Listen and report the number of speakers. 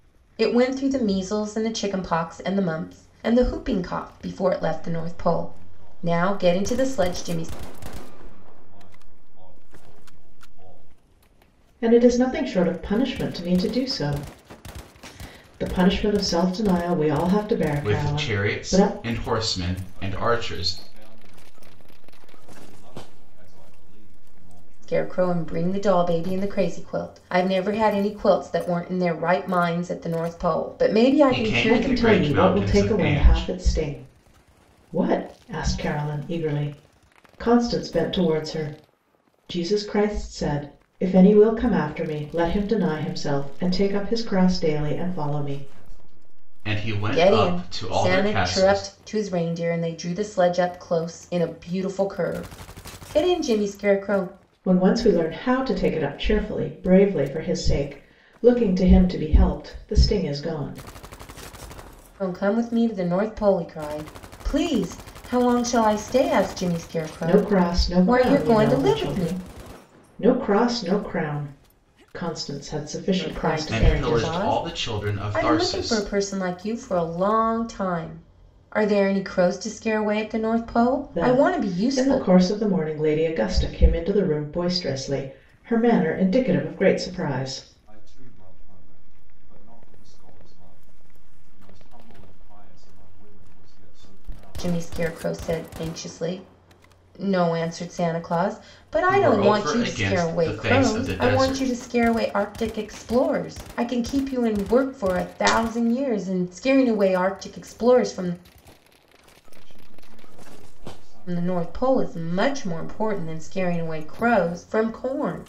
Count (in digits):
4